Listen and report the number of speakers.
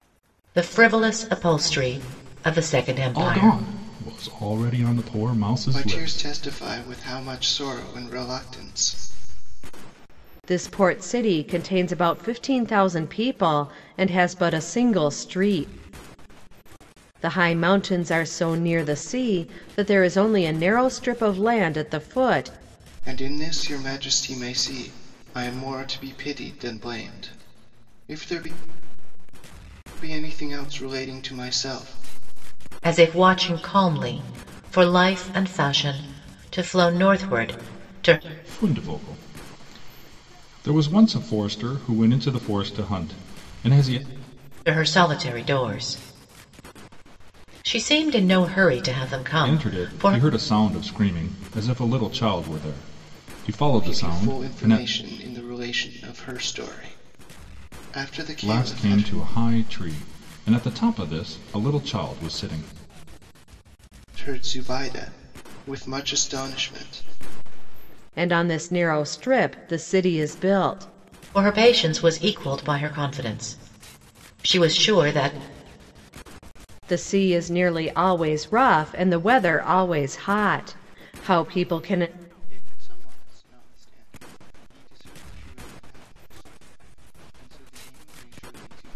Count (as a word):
four